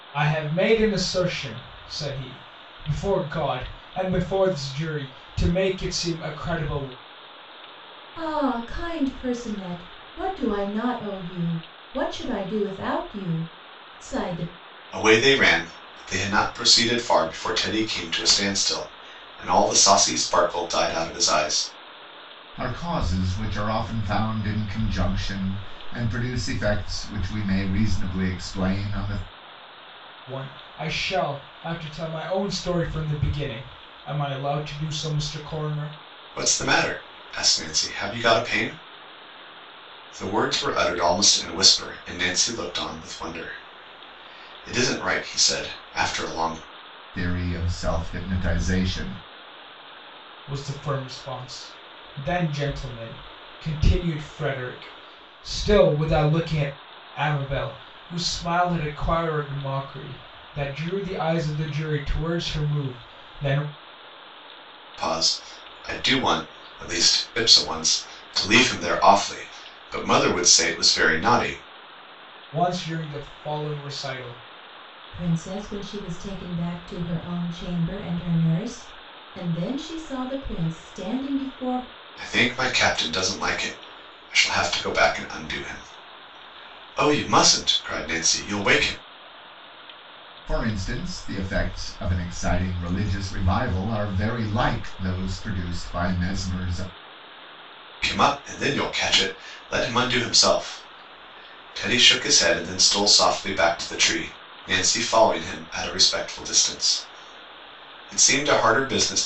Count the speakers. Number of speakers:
4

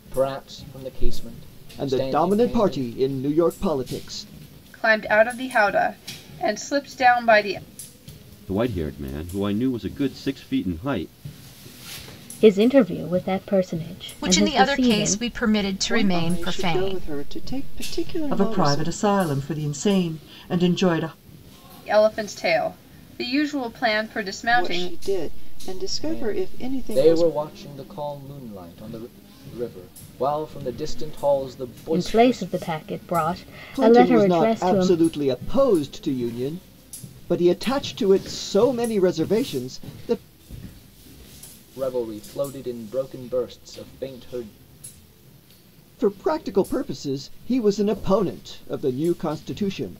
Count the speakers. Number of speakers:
8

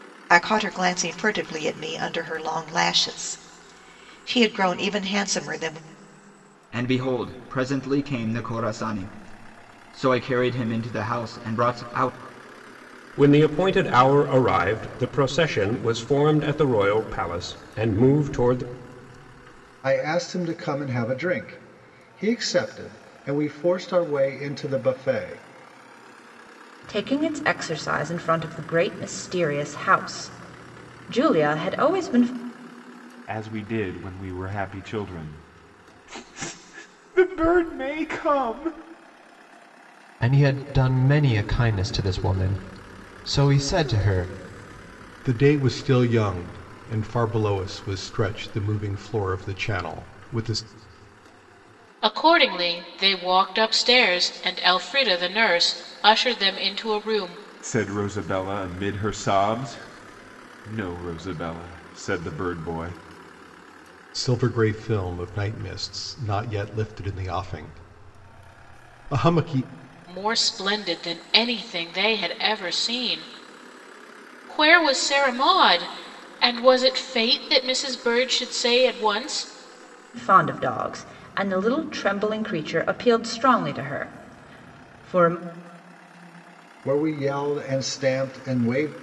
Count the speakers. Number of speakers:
9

